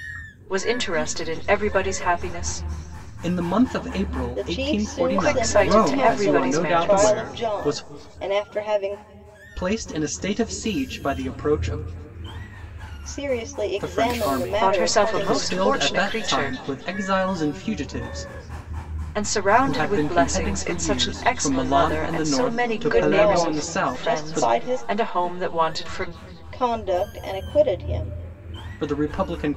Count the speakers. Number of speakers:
3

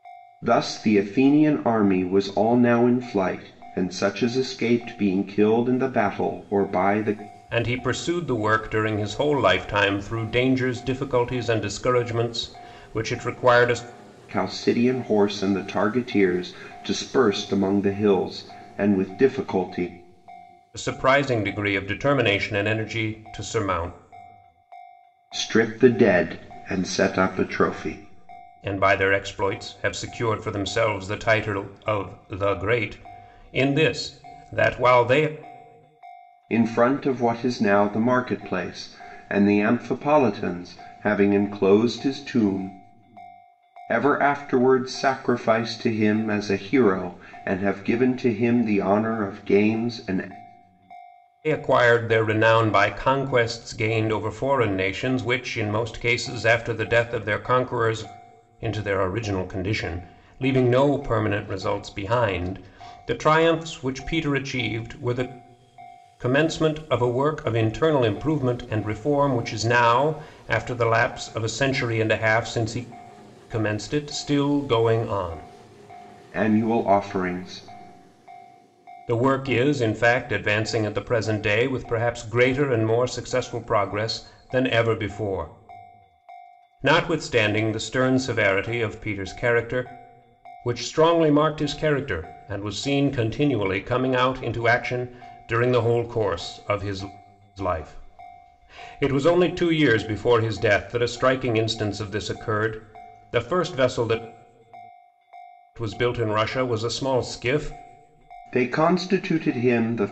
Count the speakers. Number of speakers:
2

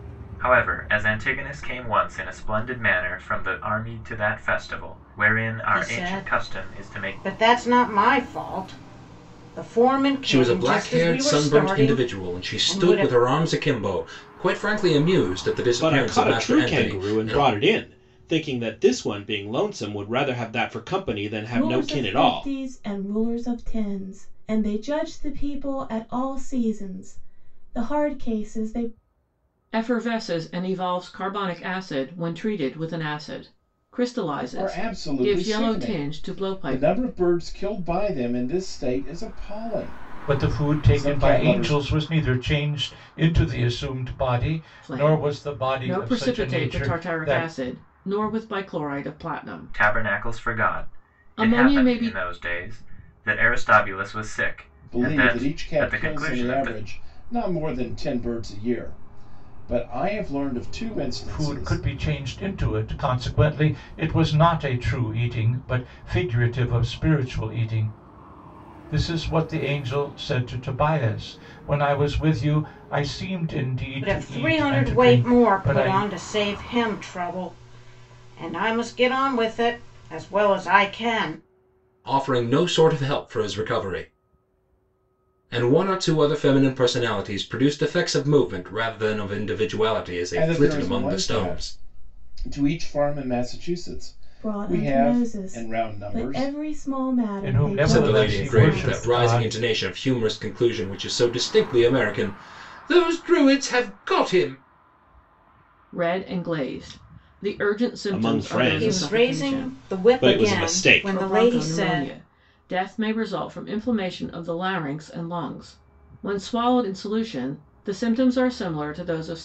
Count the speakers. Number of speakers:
8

